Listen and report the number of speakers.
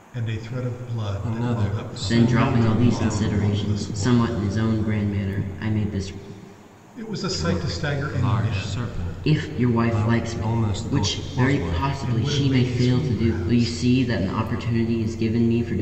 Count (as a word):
three